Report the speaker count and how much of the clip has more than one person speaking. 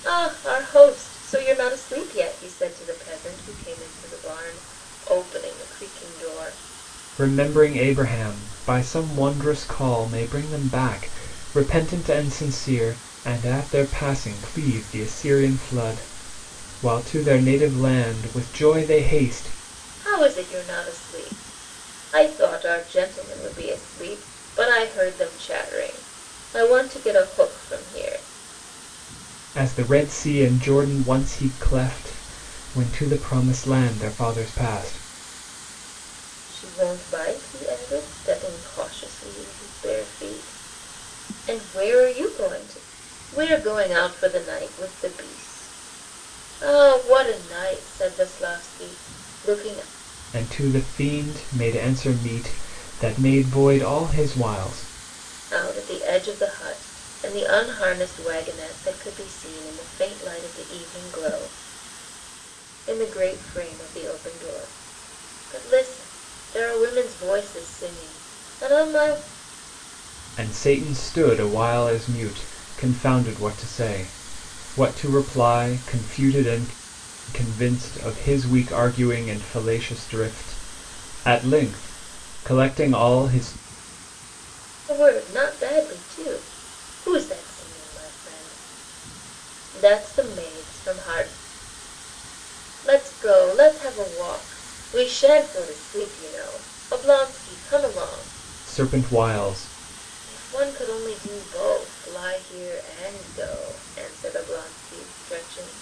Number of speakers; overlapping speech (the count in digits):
2, no overlap